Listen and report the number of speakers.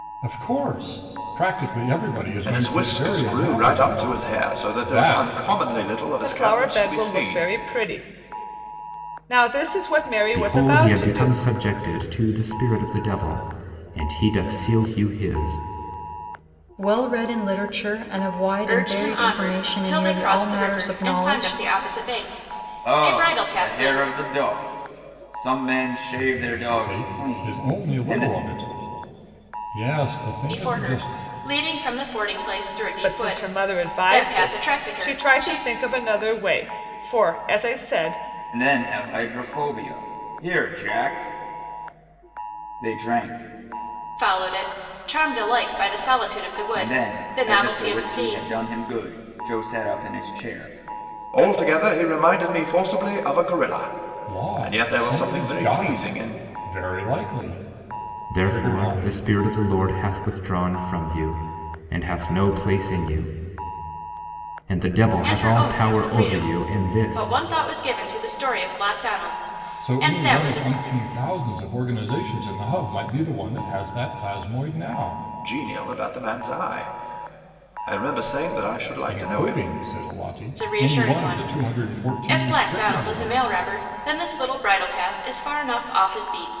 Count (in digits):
7